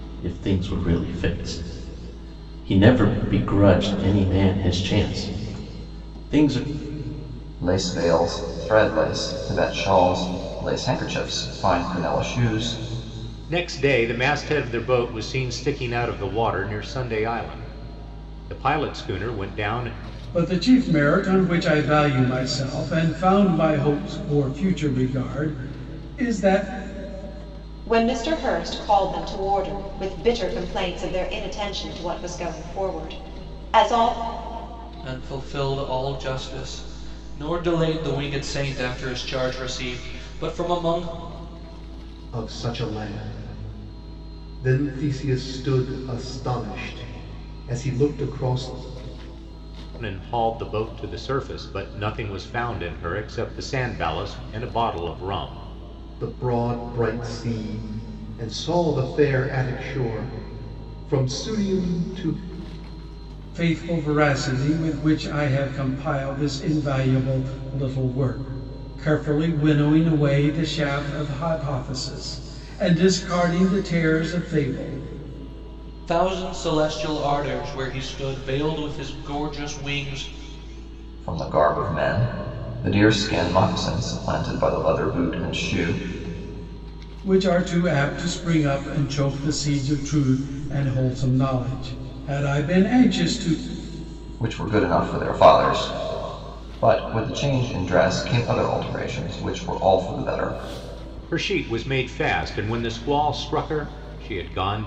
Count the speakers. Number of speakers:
7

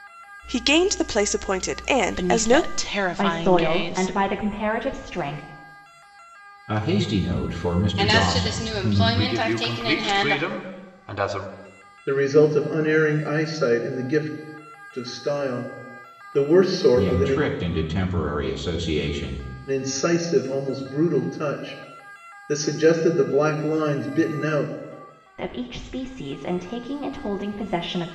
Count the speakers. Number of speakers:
7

